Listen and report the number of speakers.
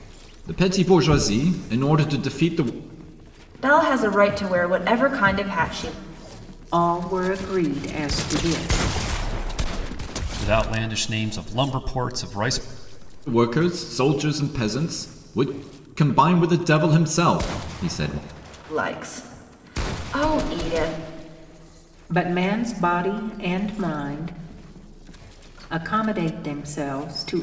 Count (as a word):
four